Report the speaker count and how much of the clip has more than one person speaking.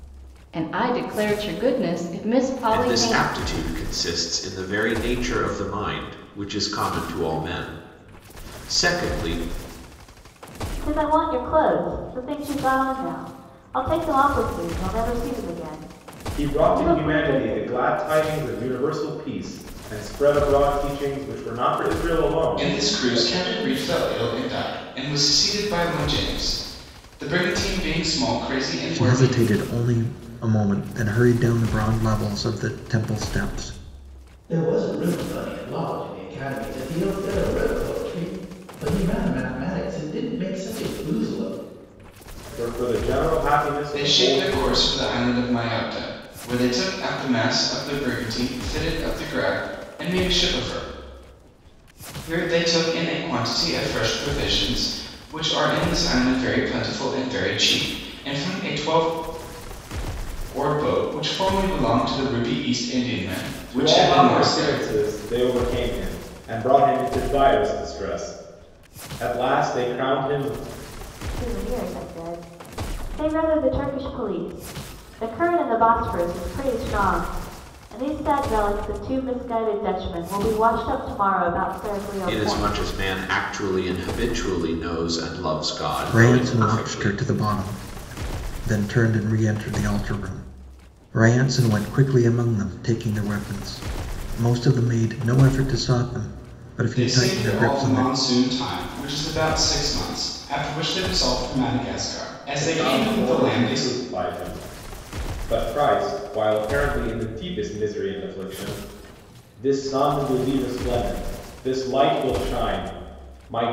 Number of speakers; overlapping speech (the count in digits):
7, about 9%